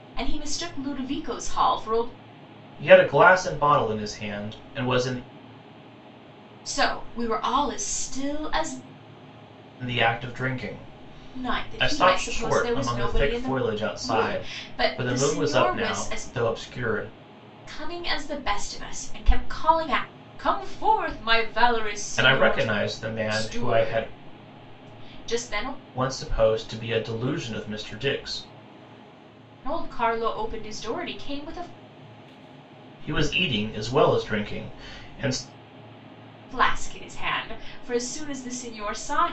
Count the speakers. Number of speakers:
2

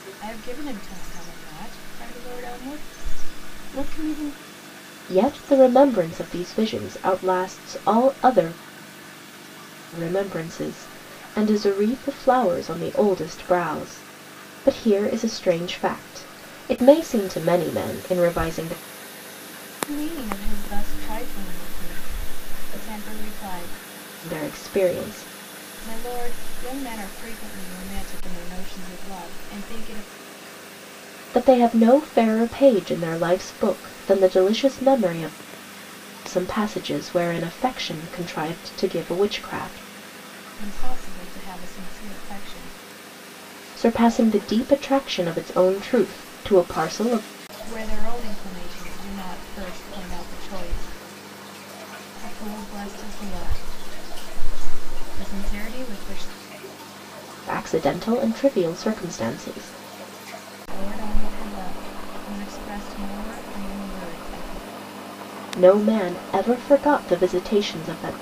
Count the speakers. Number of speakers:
2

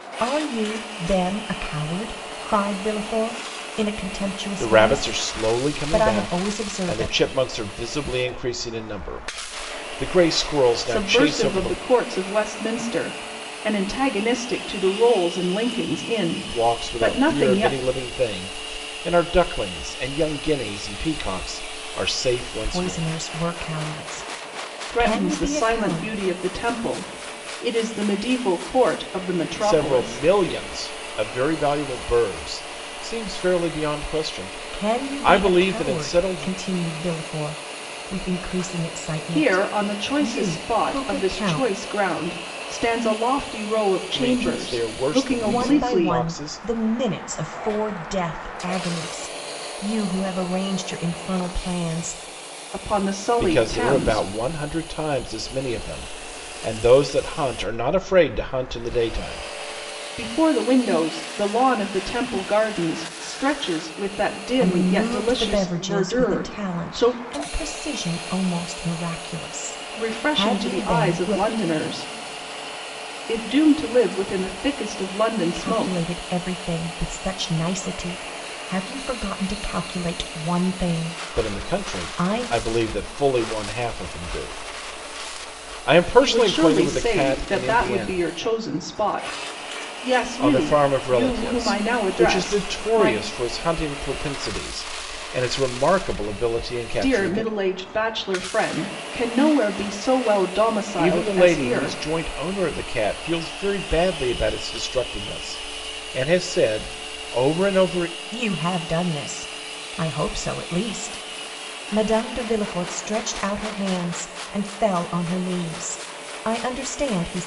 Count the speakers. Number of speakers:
3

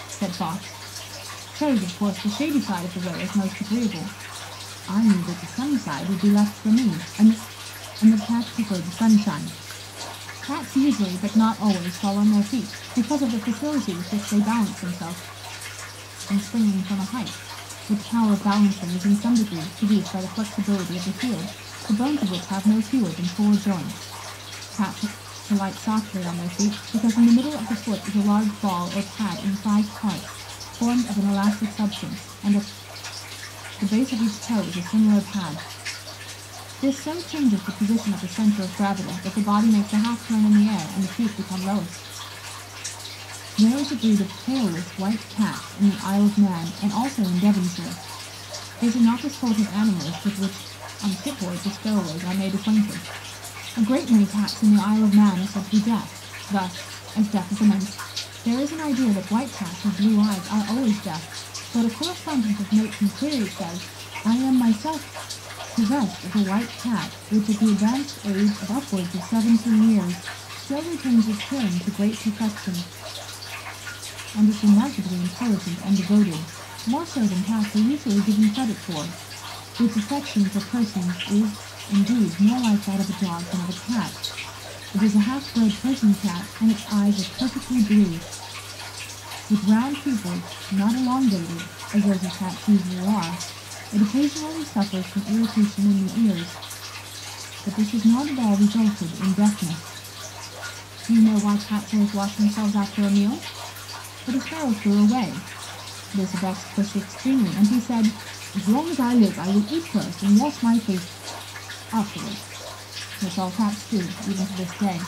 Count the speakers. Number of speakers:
1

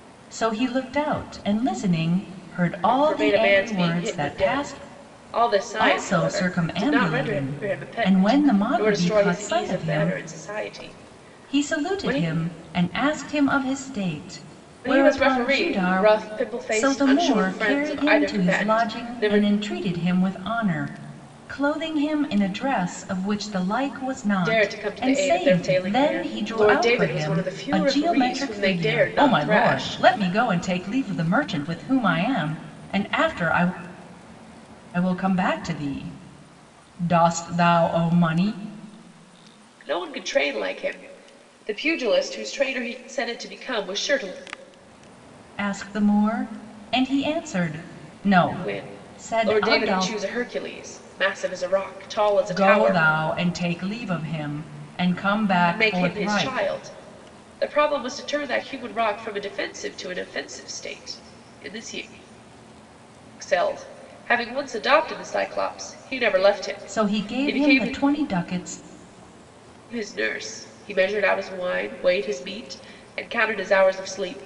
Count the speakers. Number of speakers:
2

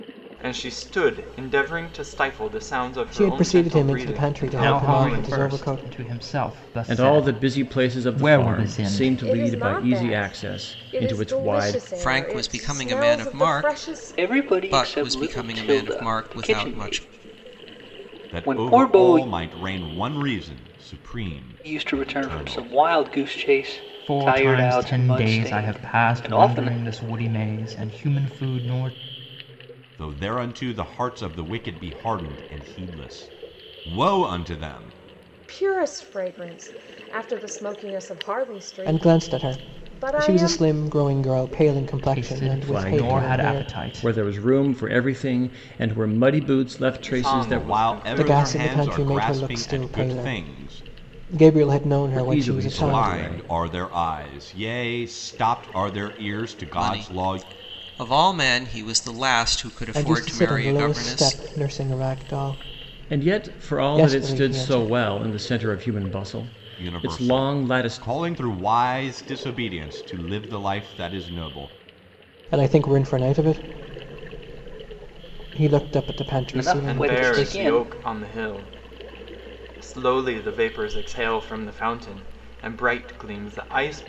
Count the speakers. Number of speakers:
8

